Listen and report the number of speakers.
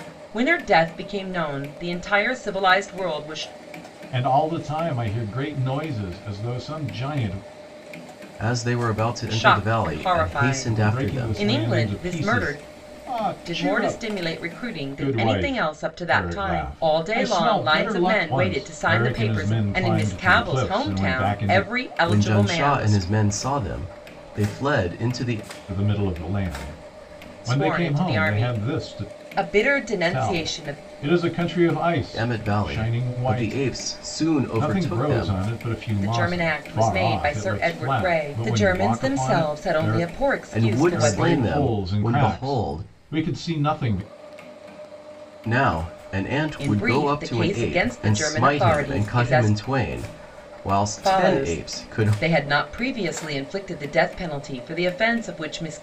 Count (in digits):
3